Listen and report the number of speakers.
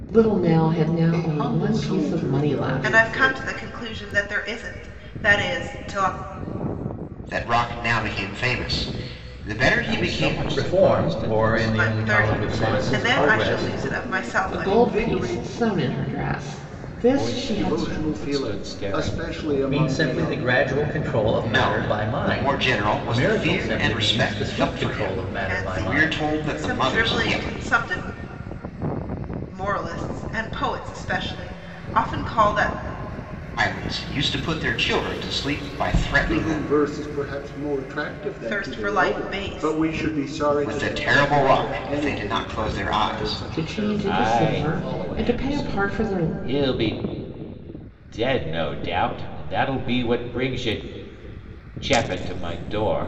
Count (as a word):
six